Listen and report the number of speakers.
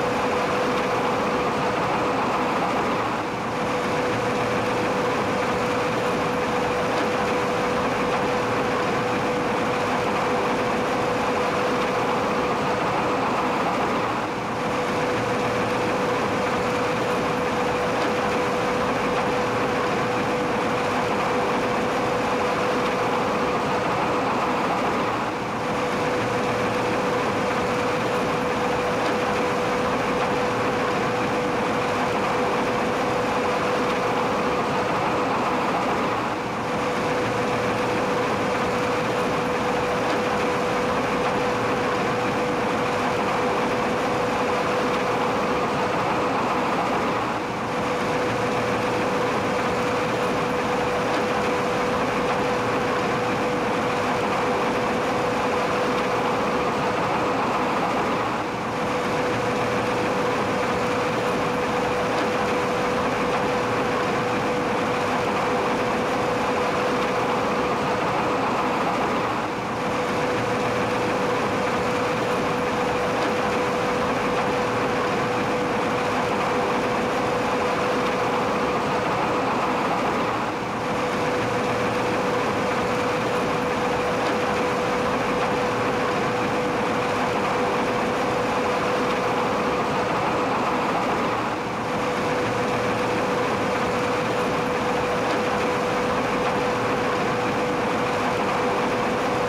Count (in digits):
0